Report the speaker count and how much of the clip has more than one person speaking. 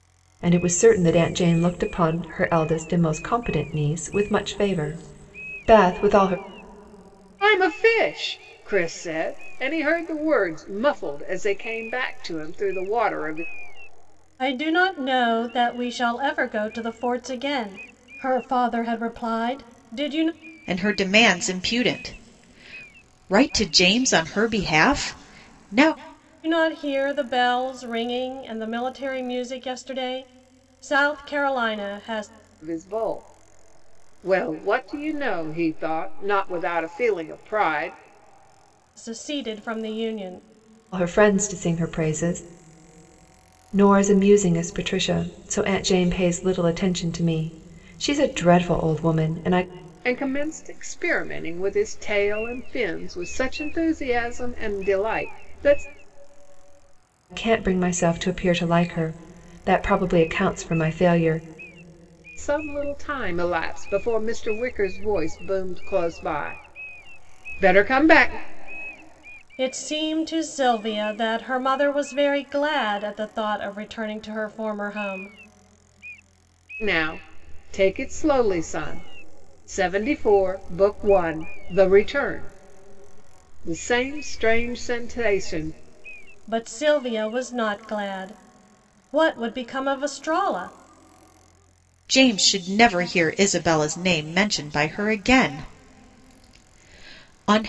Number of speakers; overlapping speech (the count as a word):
four, no overlap